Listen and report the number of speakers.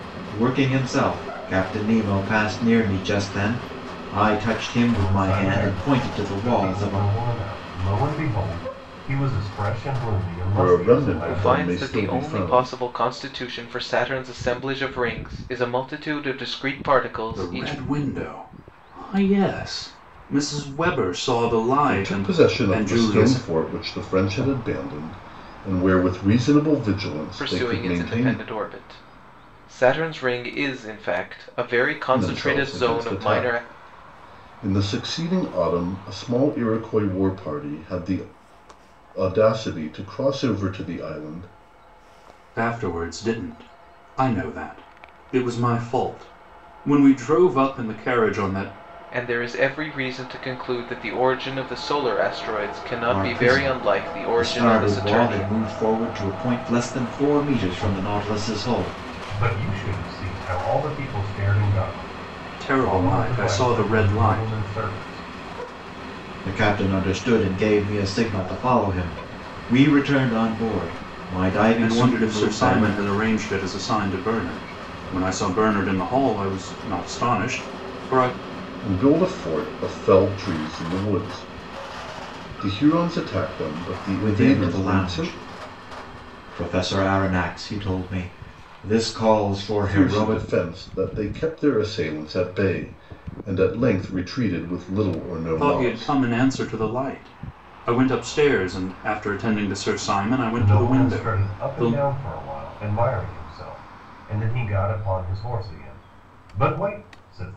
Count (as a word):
five